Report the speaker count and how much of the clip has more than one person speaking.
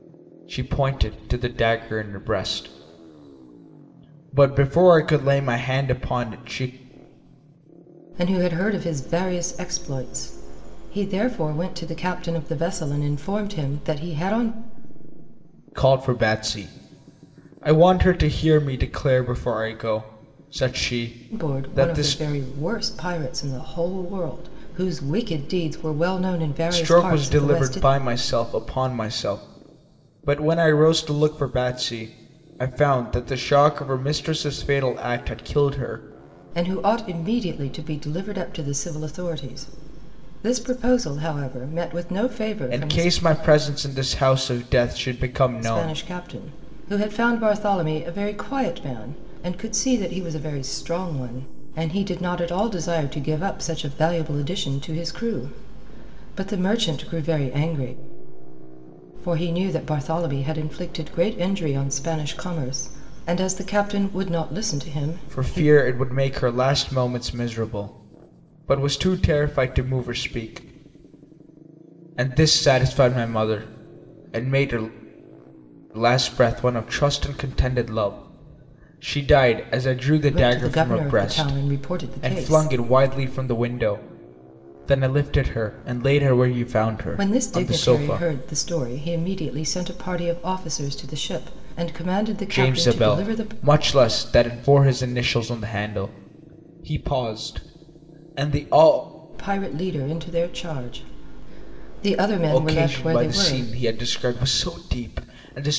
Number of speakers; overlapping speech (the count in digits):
2, about 8%